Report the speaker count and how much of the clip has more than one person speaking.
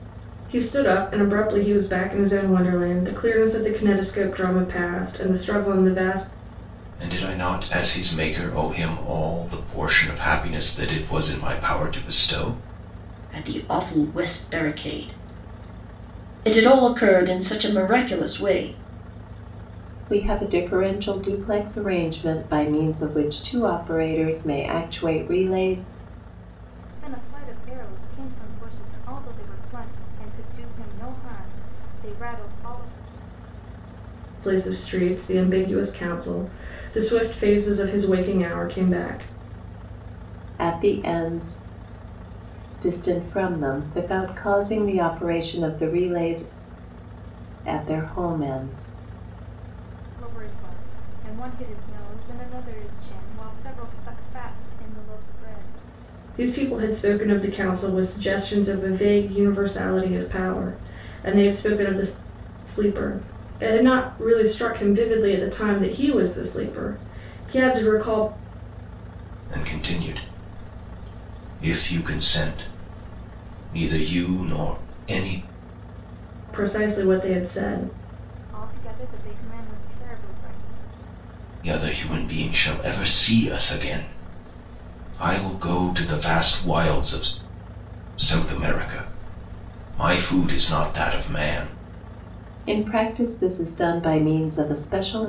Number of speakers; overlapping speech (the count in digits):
5, no overlap